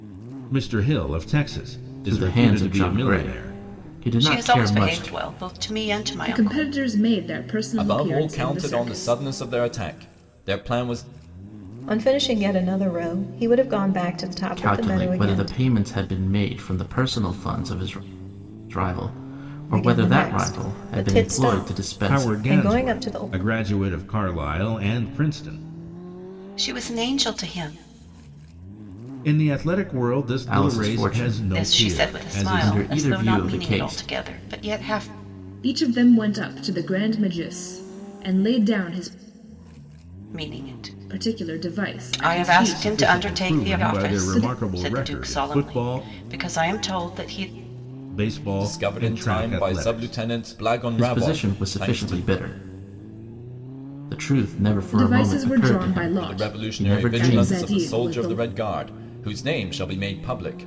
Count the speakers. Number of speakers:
six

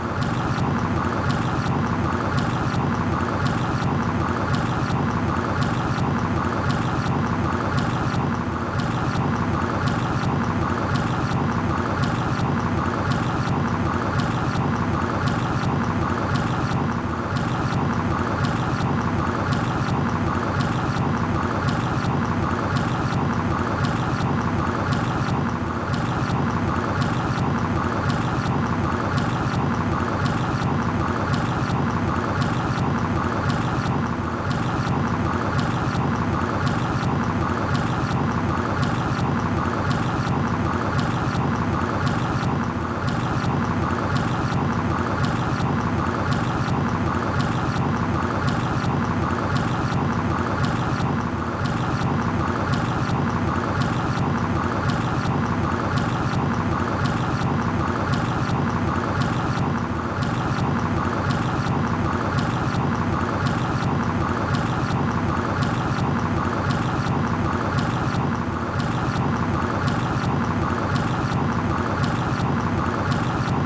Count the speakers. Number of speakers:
zero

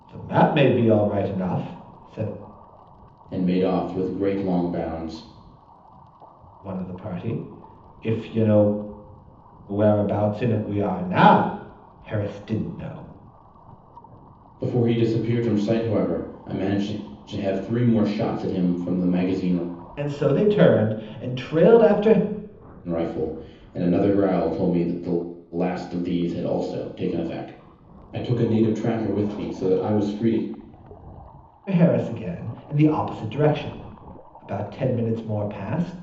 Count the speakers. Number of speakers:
two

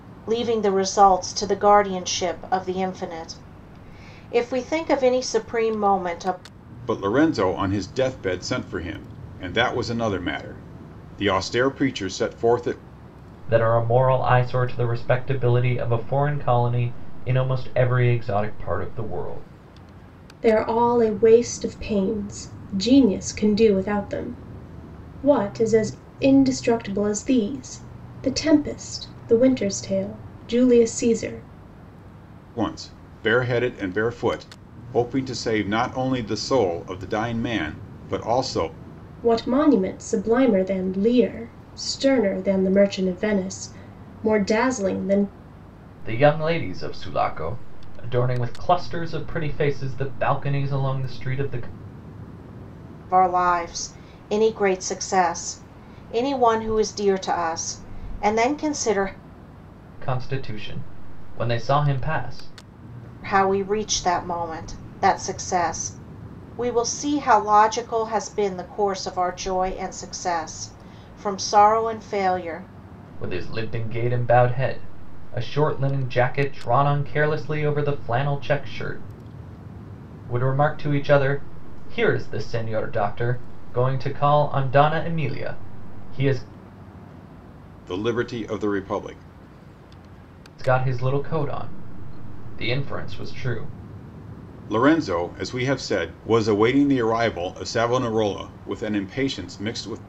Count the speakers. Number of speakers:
four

